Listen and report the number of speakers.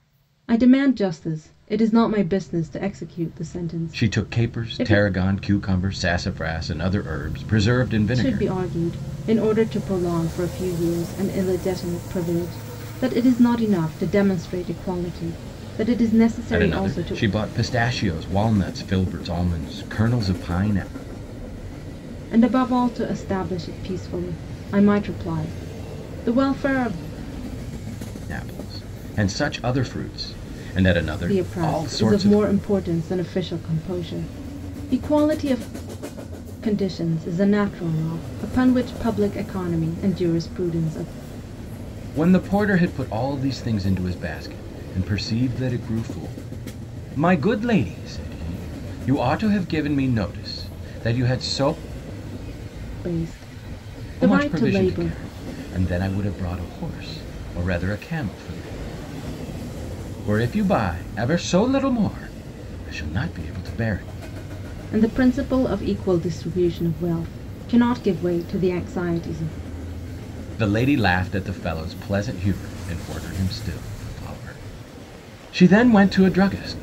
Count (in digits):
2